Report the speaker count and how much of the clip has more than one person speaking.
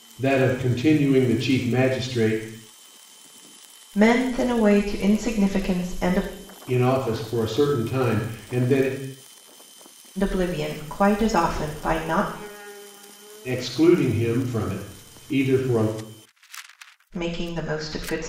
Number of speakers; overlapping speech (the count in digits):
2, no overlap